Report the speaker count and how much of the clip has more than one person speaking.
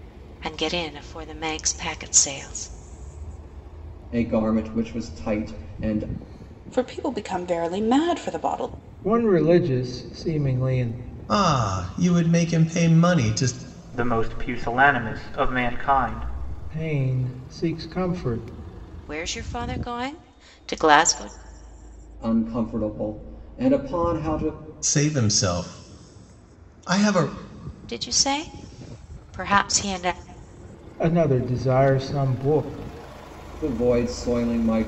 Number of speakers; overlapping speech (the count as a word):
six, no overlap